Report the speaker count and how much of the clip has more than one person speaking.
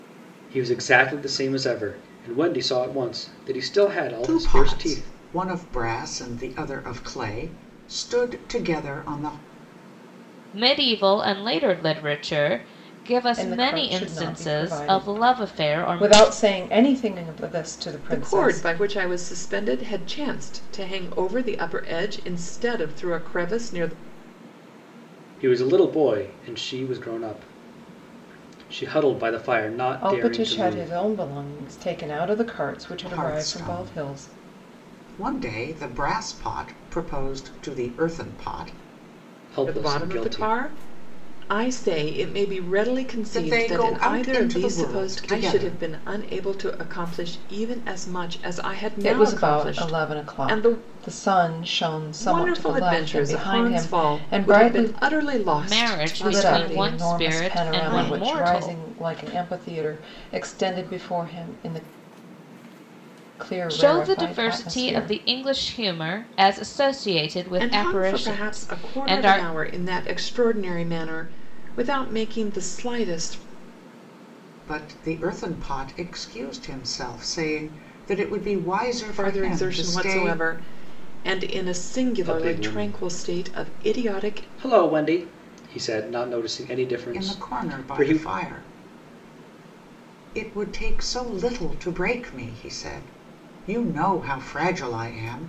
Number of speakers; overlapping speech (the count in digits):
5, about 27%